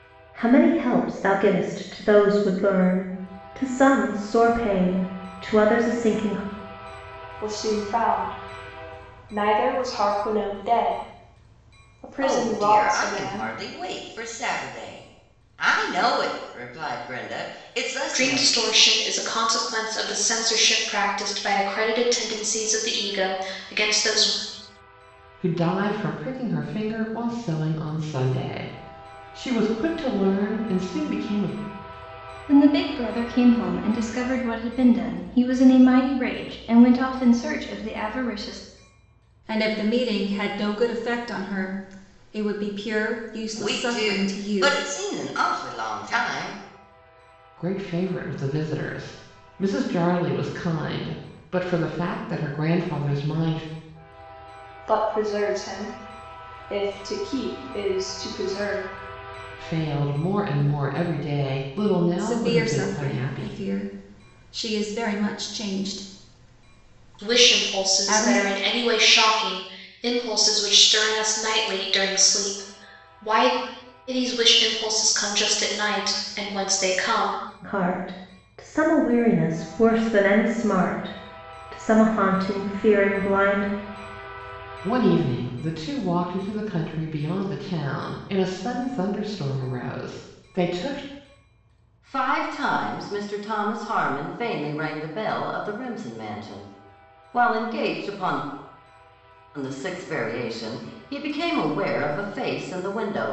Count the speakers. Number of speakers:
seven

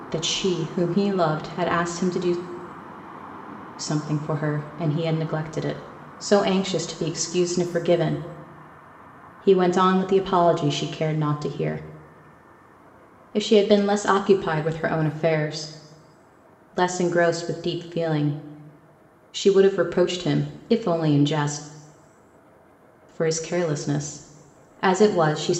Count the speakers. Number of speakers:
one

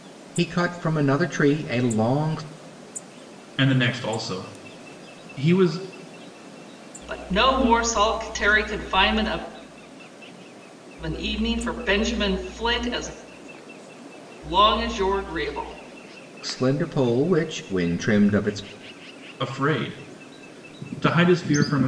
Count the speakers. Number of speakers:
three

